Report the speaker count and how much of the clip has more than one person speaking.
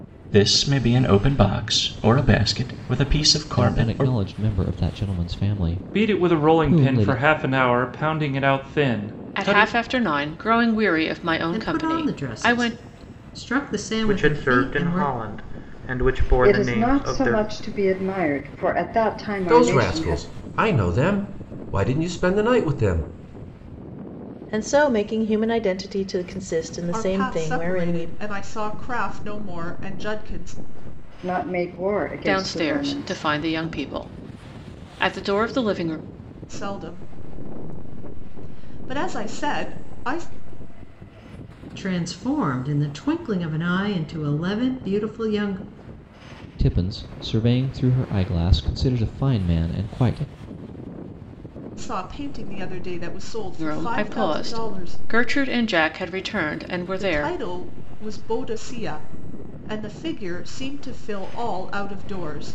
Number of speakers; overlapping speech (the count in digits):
10, about 18%